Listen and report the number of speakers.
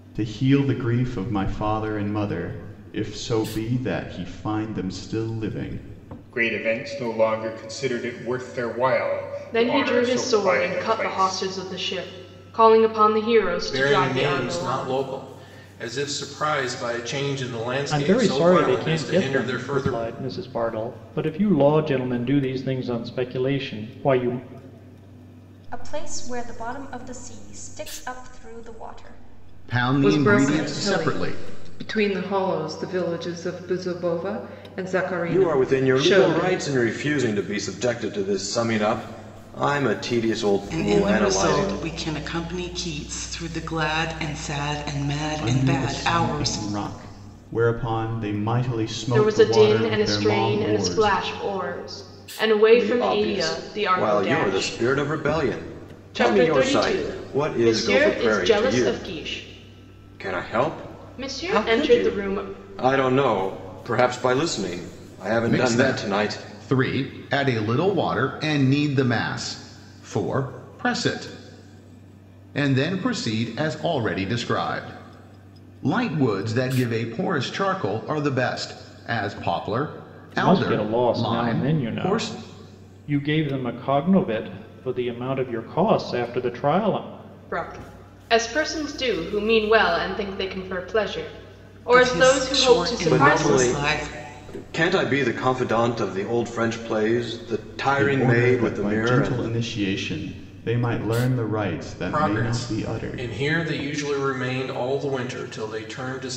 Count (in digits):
10